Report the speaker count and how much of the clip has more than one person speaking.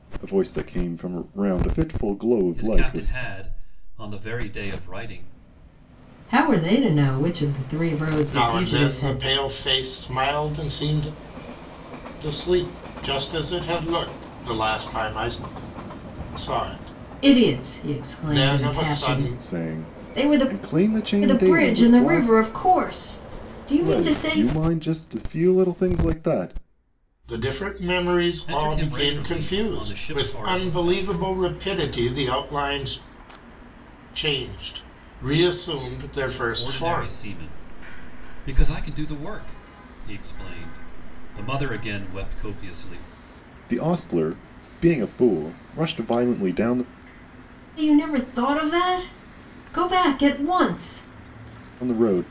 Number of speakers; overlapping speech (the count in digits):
4, about 19%